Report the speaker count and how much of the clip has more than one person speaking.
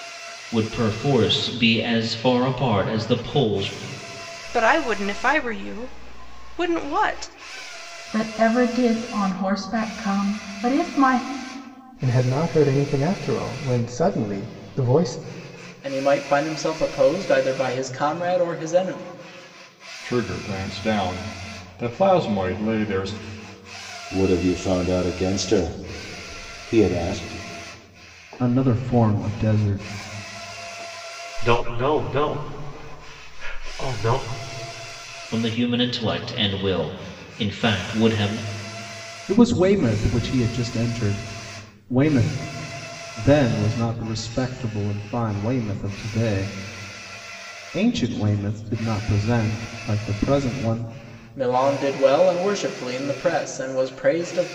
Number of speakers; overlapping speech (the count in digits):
9, no overlap